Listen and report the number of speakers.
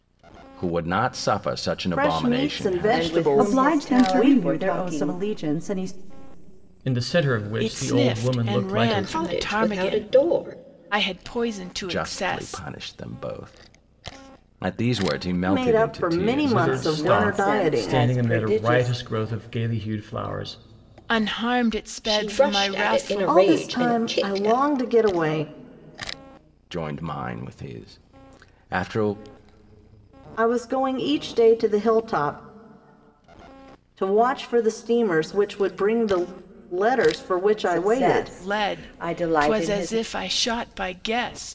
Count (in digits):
7